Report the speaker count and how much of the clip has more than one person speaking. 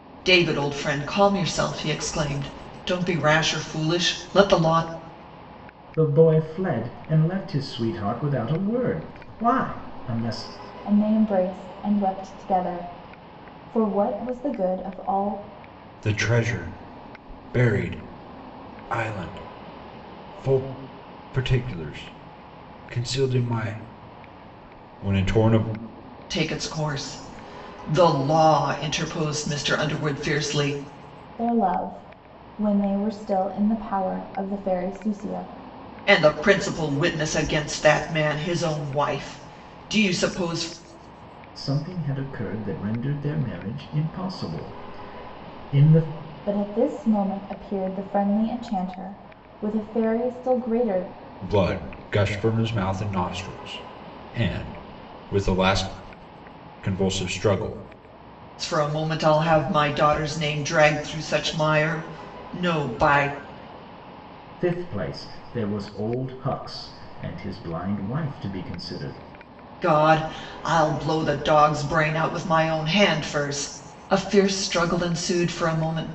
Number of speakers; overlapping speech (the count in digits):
4, no overlap